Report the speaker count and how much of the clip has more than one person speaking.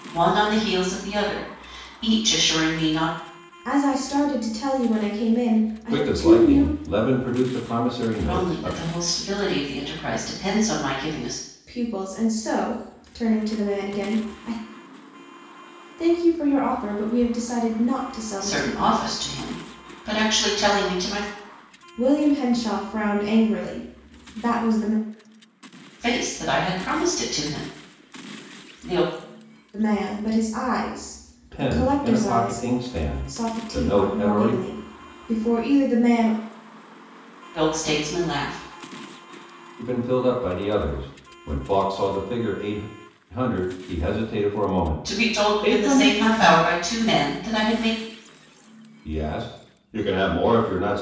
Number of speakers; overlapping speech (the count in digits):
3, about 11%